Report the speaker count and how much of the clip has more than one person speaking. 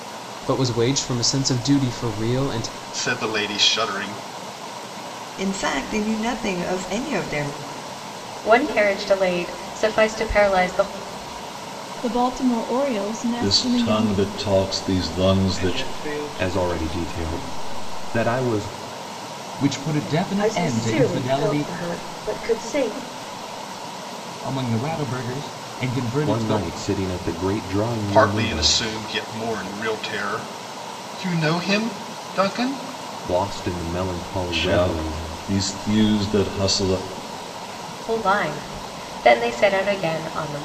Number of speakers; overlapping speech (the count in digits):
10, about 14%